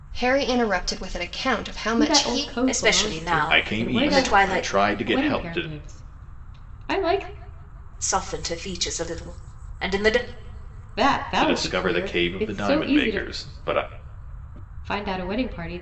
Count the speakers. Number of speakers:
4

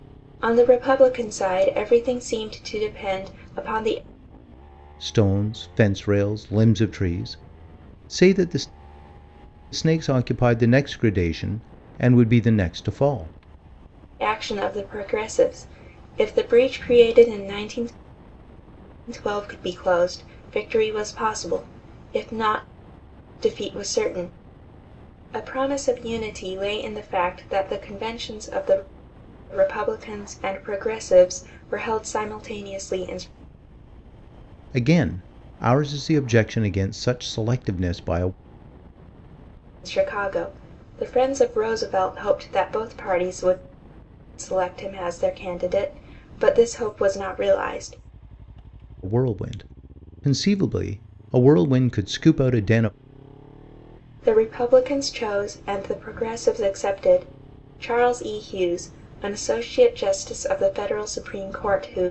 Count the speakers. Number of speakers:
2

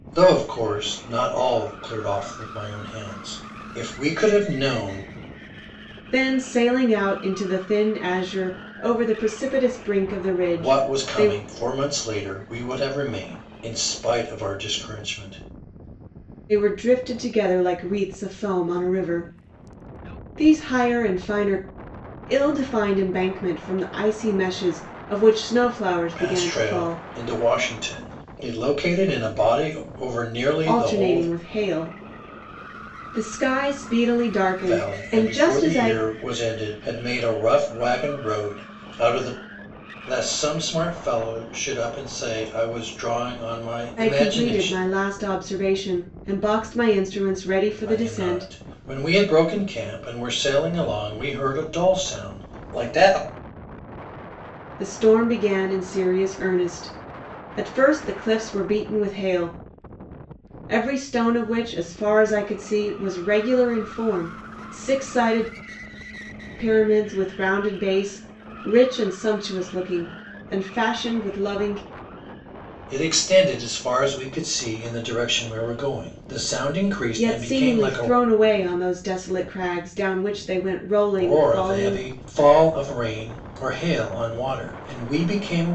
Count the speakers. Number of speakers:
2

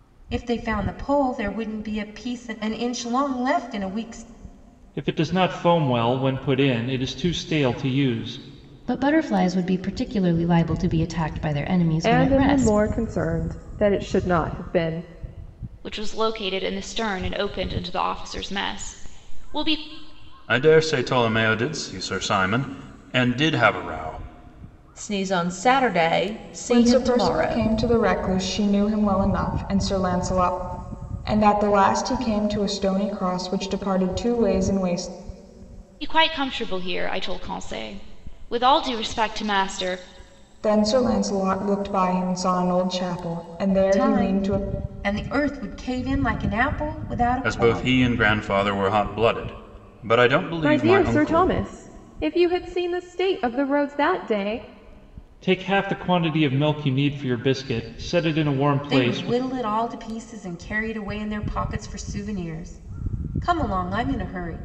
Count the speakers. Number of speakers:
8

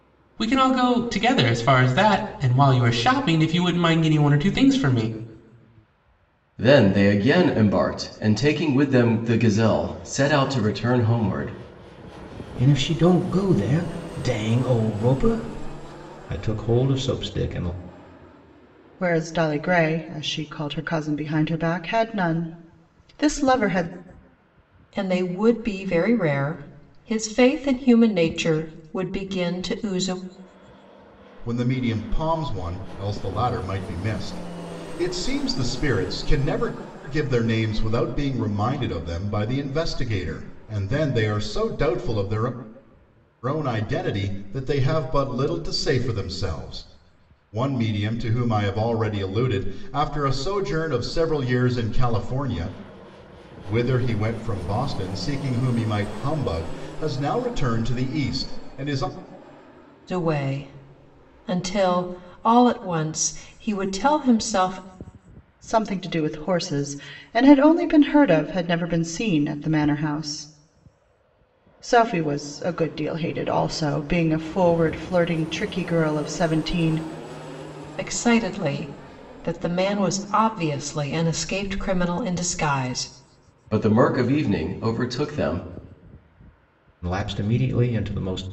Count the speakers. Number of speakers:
6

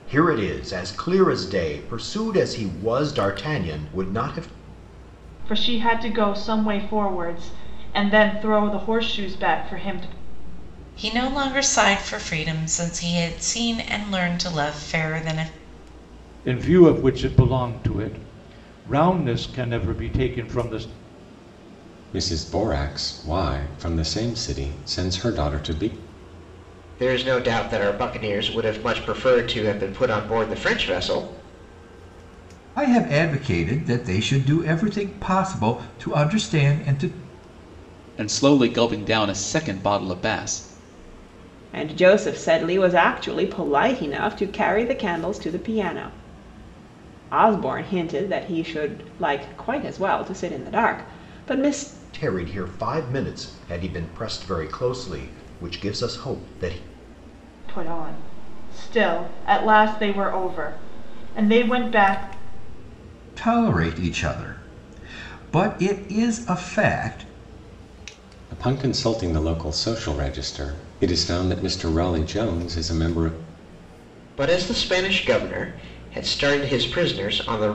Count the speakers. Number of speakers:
9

